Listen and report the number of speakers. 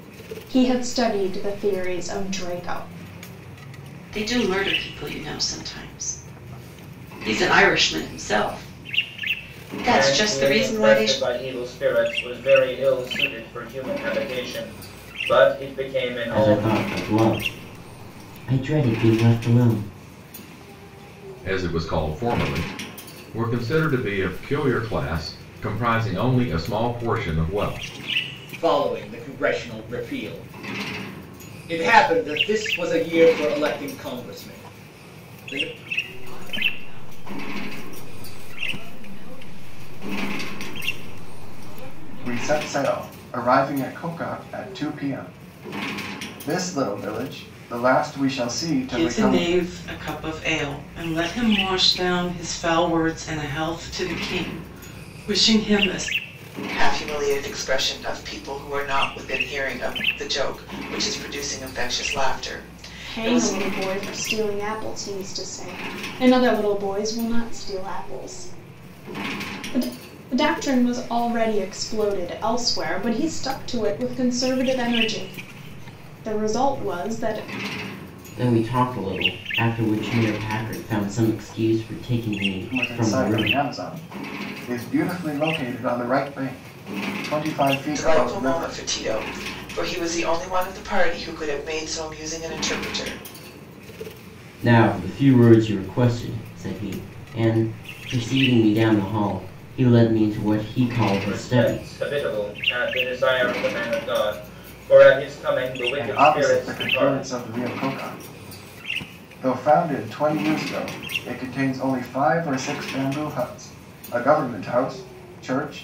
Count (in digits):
10